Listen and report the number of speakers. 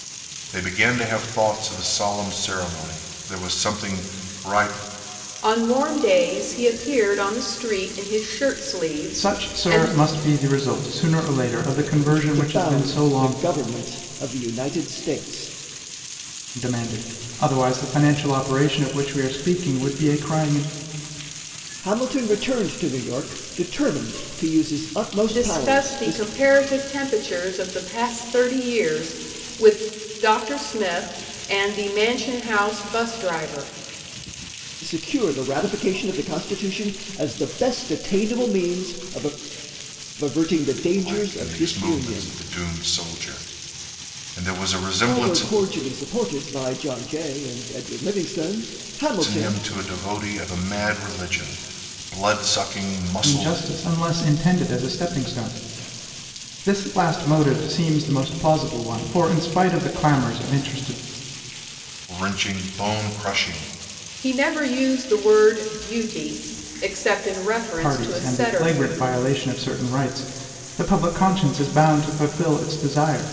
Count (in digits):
4